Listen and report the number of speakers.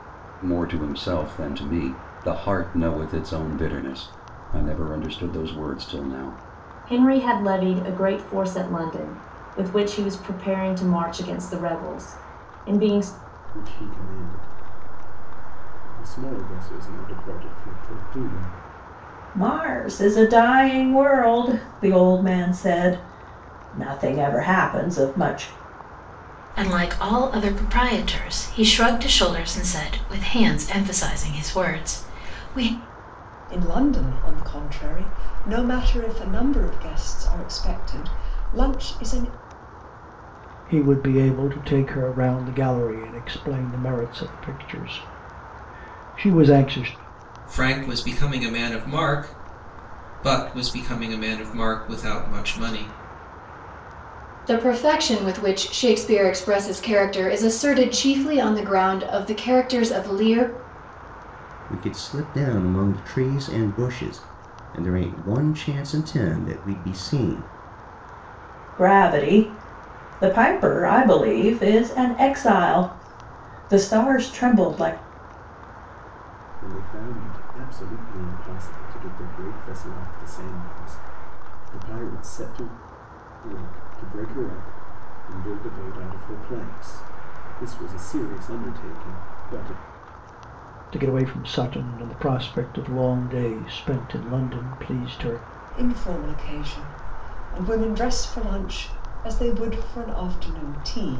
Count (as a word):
ten